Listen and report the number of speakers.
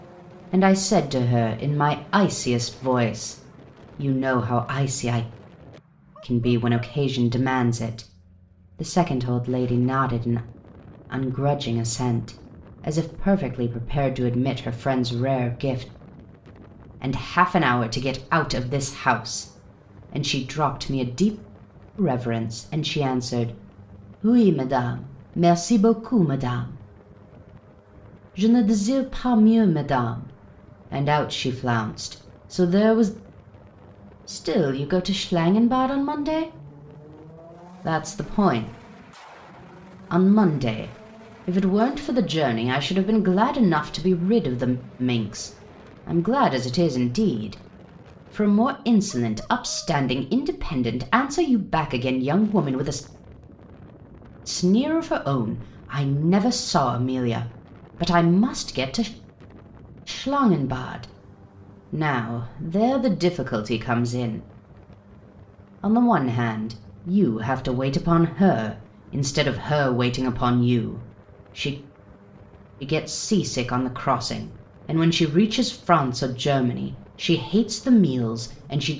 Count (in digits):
1